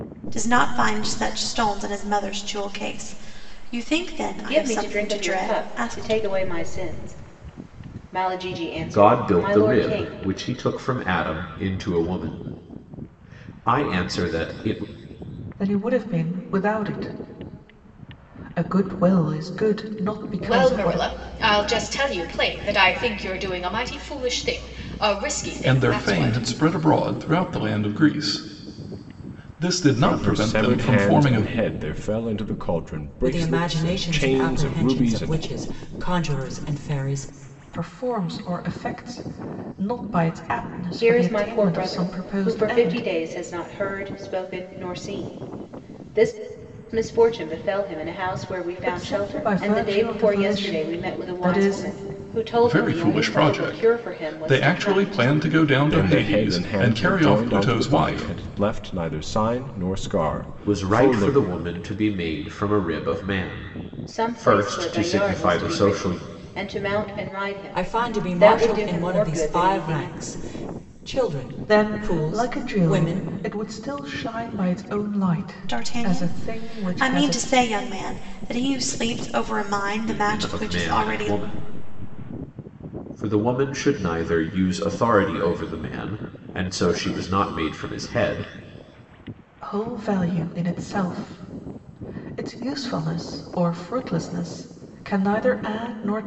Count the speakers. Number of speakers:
eight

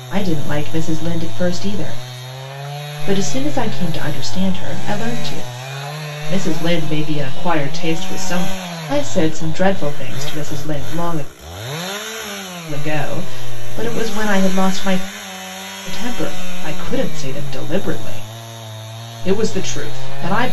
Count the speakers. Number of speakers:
one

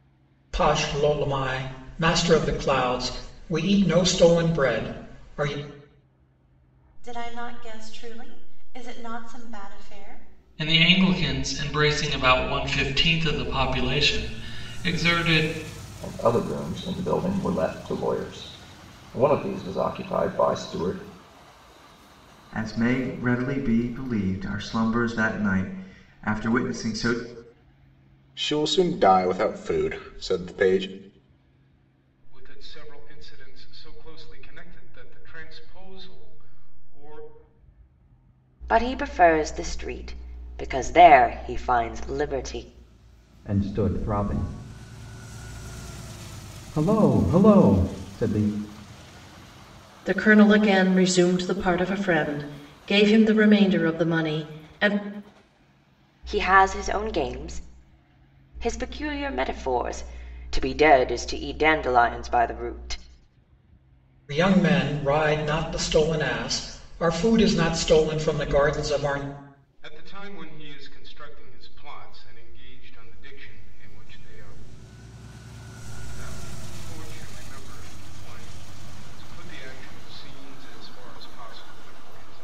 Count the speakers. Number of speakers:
ten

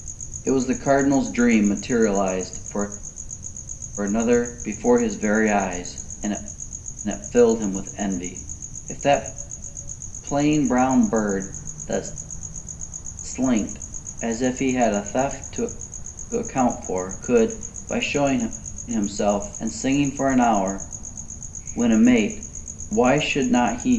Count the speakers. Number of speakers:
one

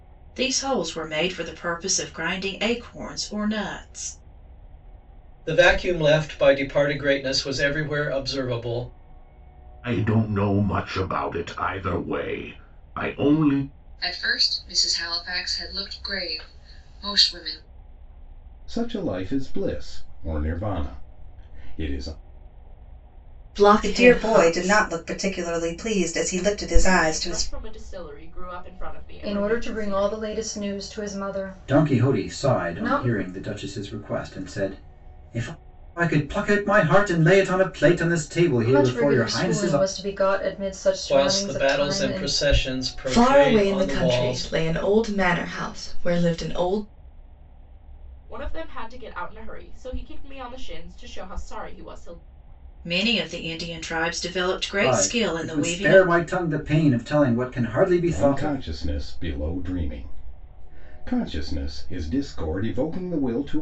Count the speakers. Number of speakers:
ten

